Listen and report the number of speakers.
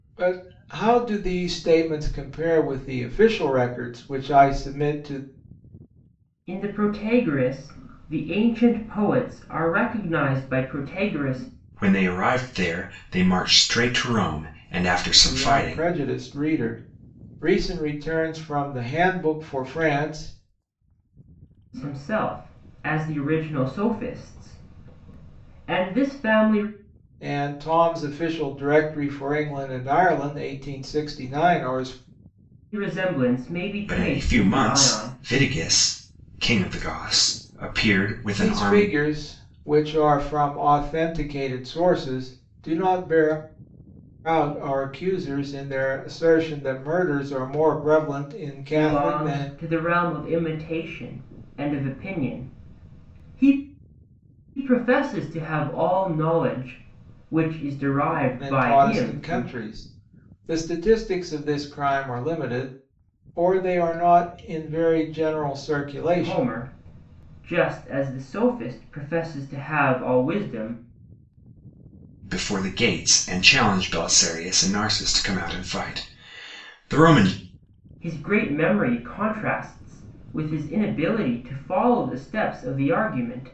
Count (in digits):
3